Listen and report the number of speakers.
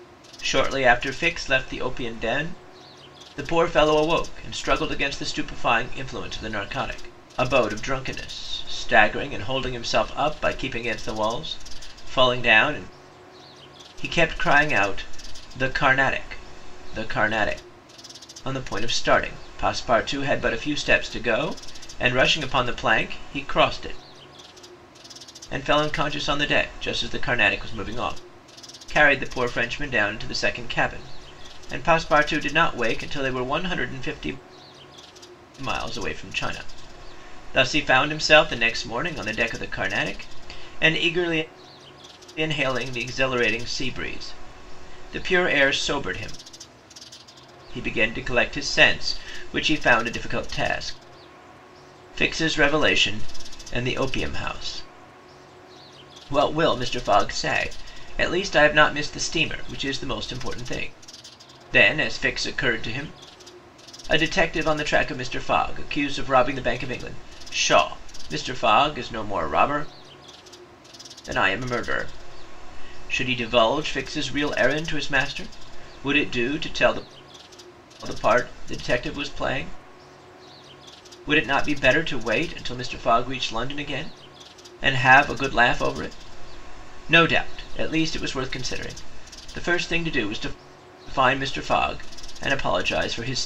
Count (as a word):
one